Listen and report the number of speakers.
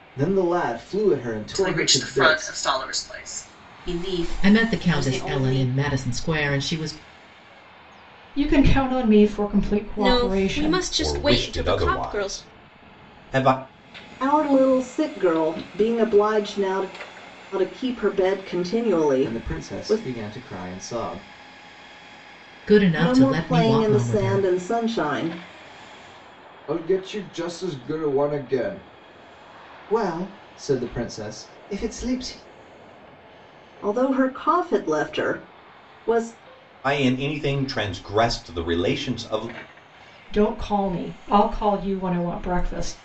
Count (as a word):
eight